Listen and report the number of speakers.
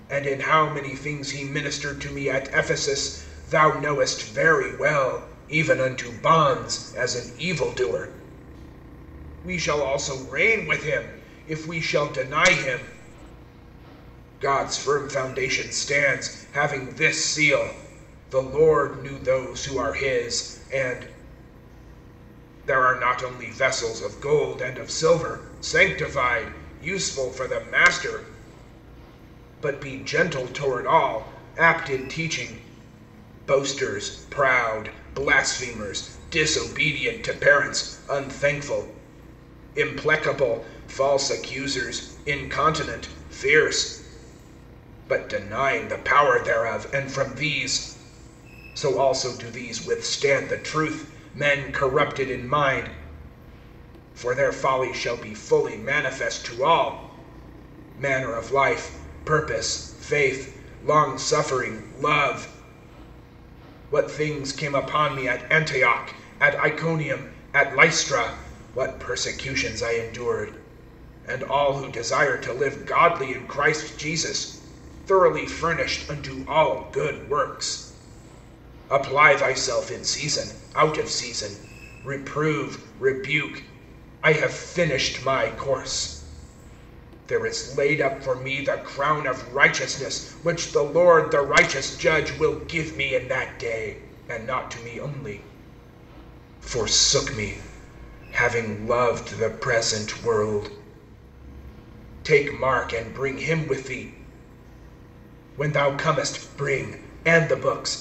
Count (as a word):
one